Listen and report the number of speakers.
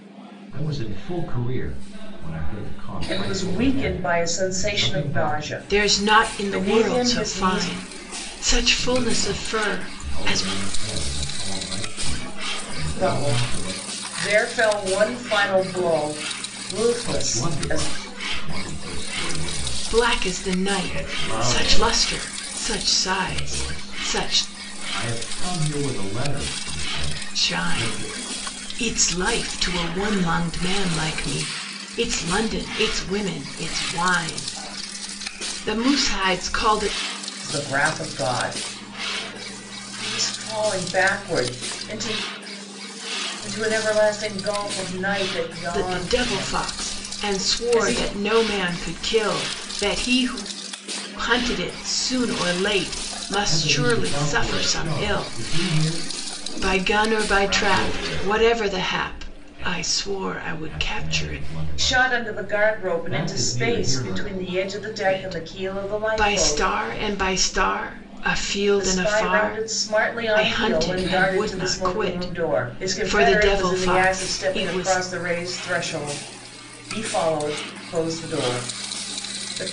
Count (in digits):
3